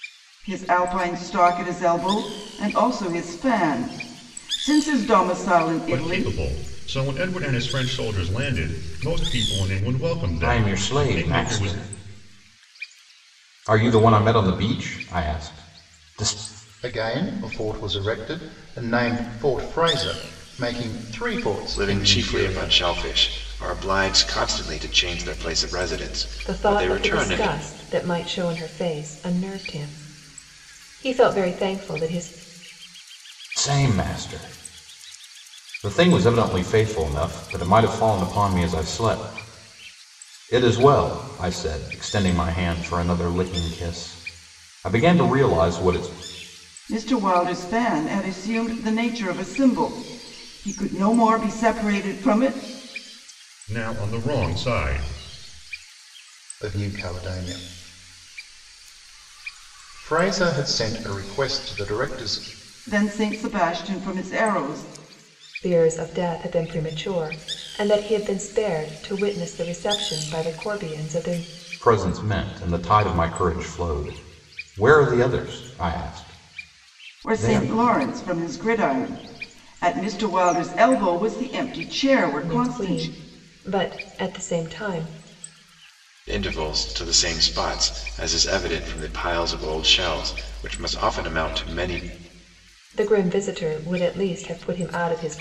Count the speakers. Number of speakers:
6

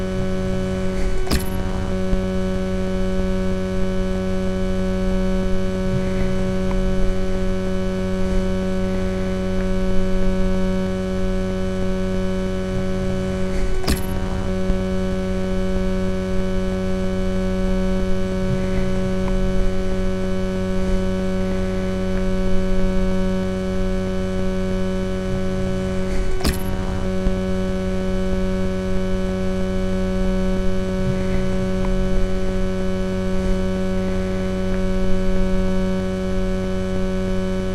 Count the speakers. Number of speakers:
0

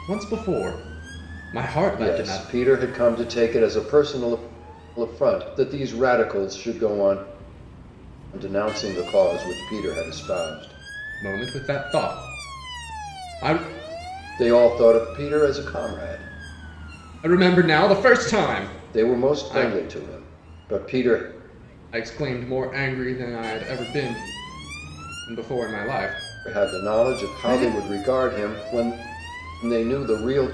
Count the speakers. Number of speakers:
2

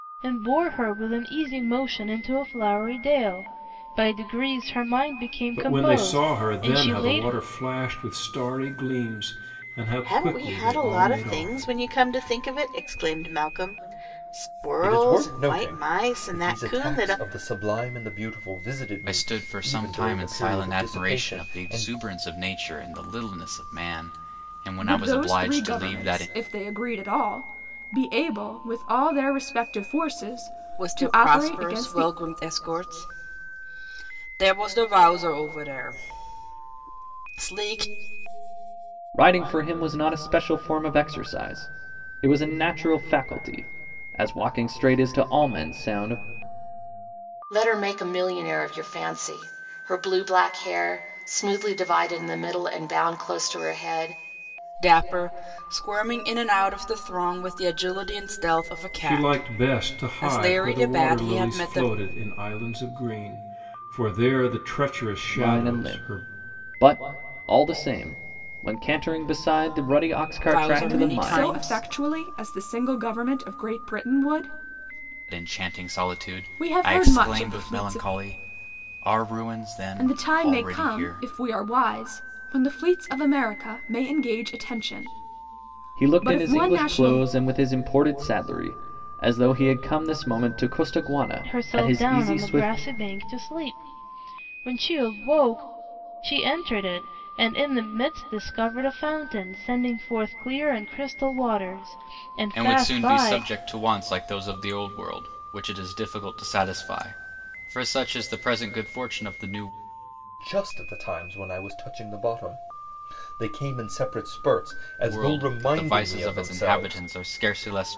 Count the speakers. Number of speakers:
9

